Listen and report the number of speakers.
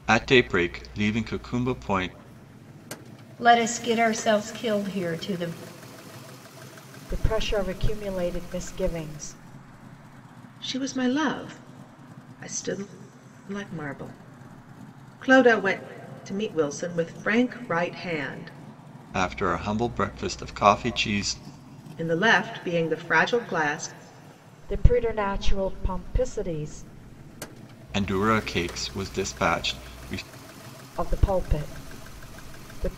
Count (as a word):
four